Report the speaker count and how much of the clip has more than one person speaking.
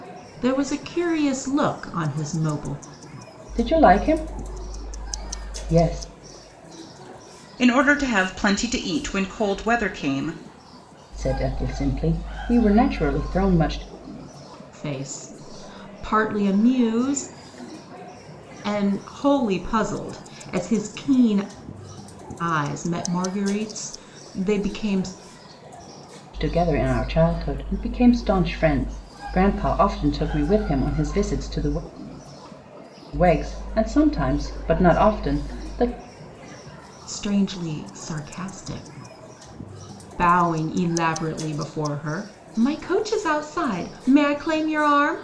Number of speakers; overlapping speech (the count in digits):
3, no overlap